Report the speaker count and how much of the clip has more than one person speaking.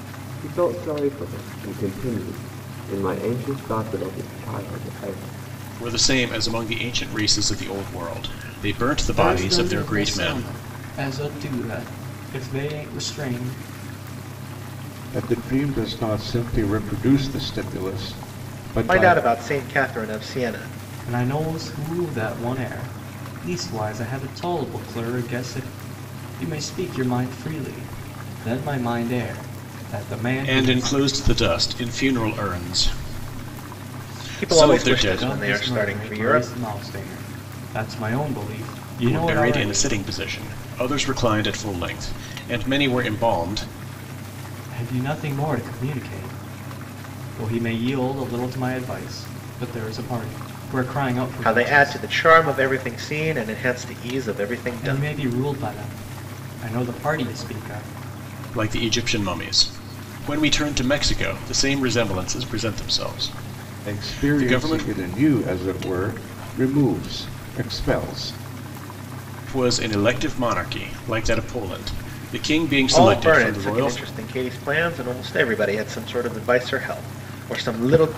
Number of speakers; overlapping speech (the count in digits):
5, about 11%